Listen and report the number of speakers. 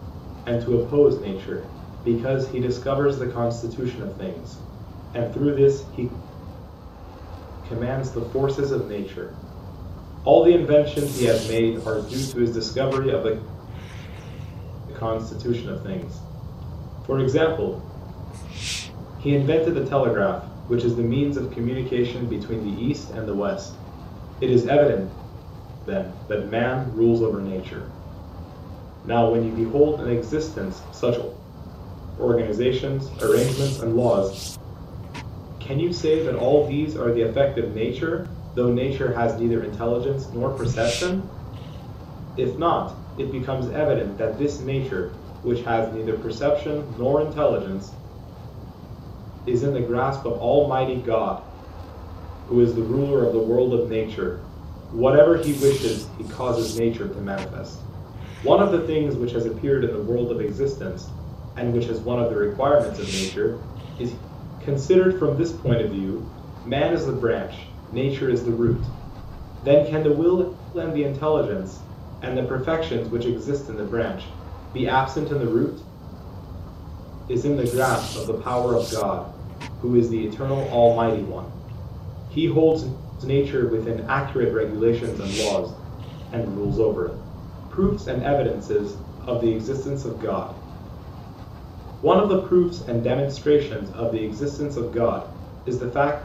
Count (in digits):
1